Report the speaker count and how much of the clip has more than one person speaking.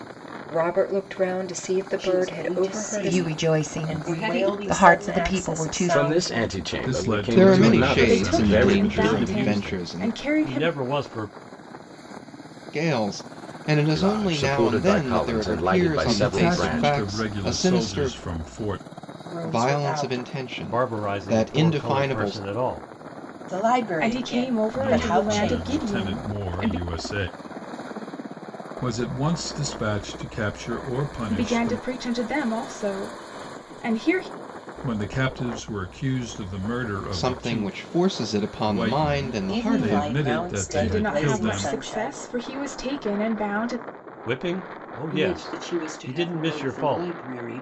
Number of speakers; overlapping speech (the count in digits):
9, about 52%